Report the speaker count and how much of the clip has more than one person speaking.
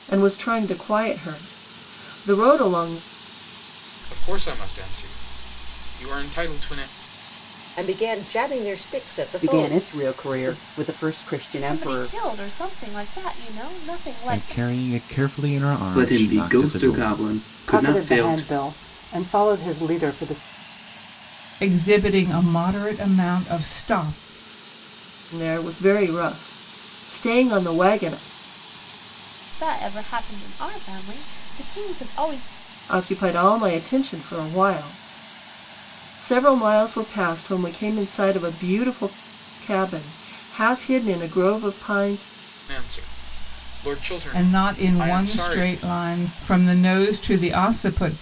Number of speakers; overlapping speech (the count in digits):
9, about 12%